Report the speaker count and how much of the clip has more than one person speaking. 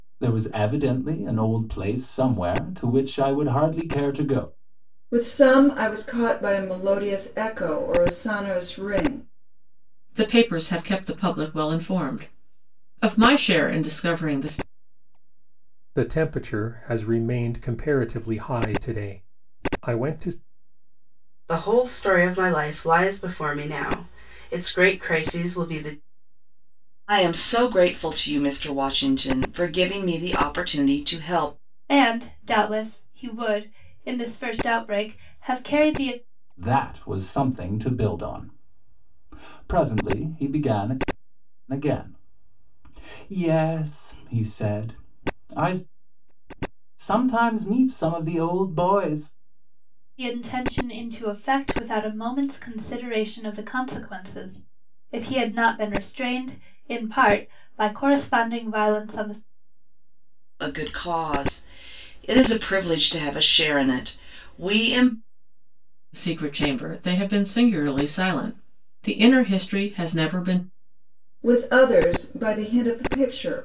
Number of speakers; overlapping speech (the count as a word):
seven, no overlap